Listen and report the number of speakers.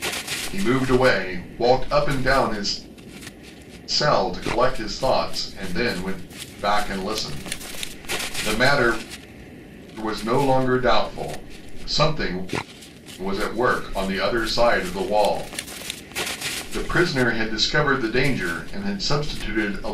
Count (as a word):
one